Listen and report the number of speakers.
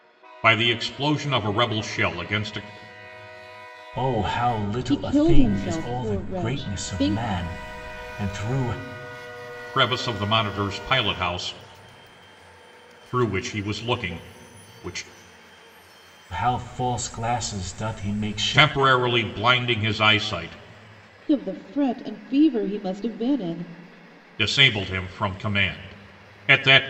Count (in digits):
3